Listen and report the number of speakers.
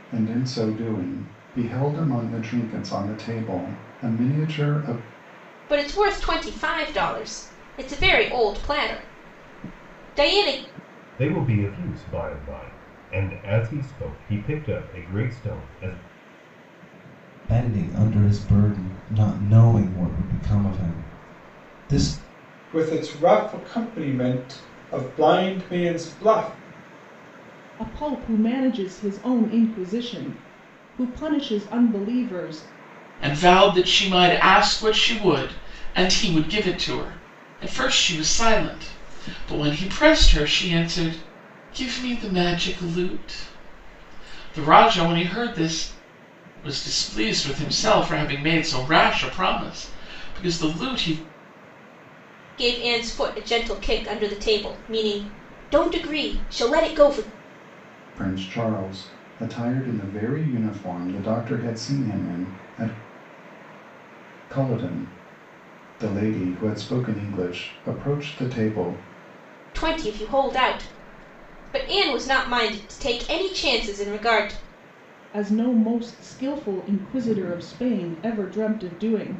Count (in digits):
7